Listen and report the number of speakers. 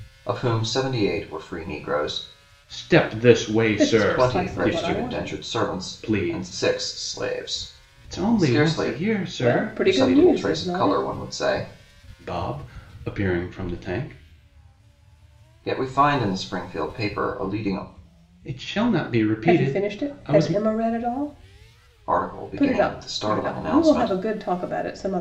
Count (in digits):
3